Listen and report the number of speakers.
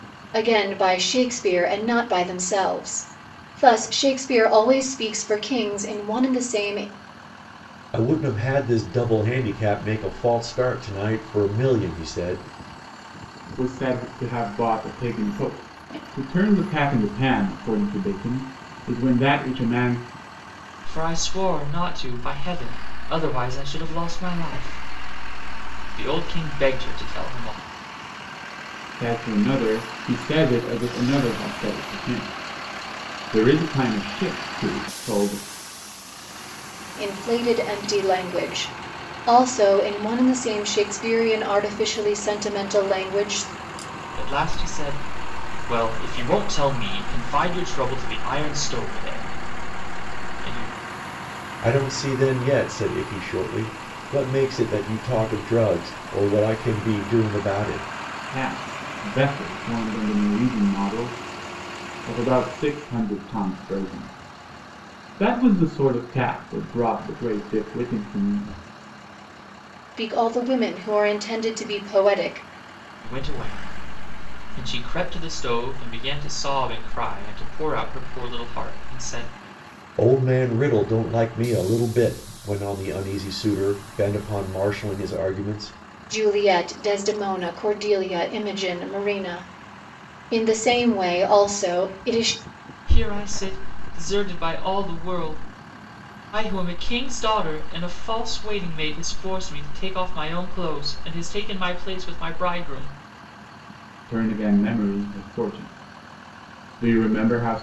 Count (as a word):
four